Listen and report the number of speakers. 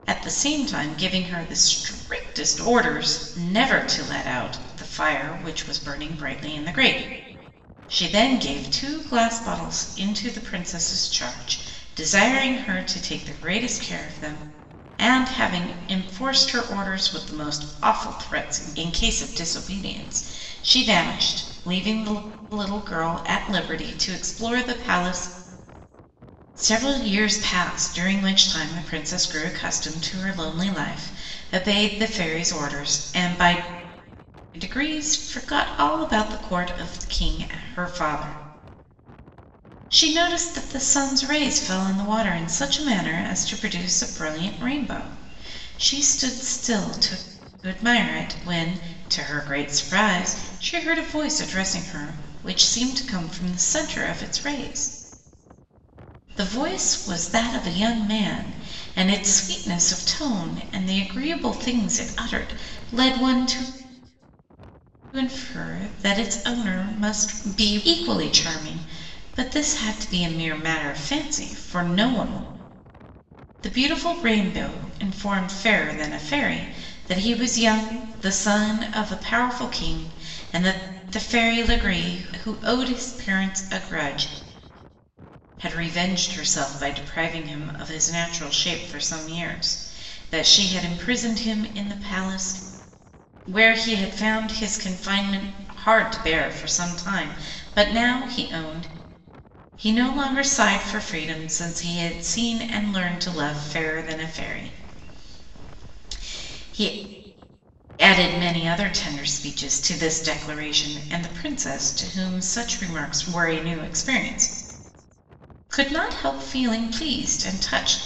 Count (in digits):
1